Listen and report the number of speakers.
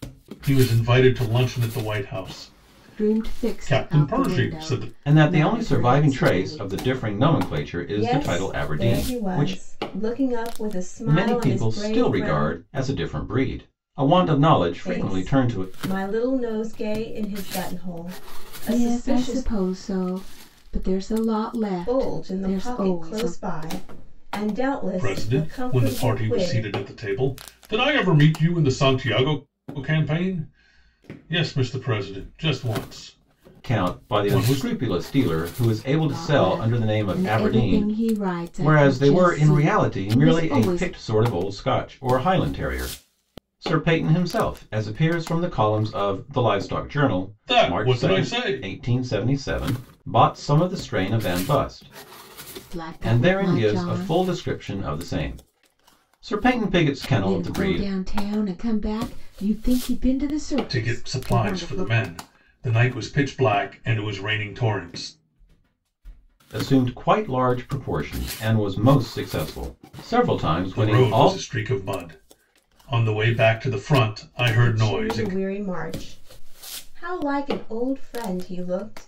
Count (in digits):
4